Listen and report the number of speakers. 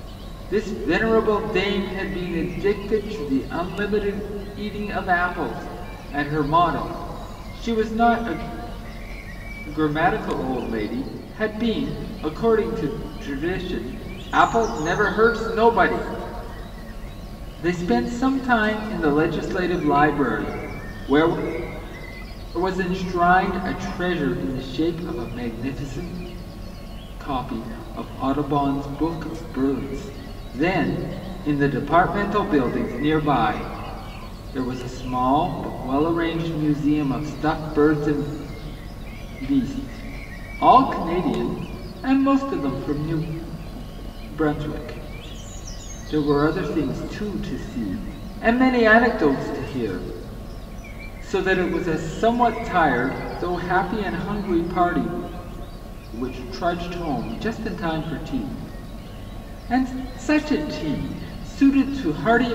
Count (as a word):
one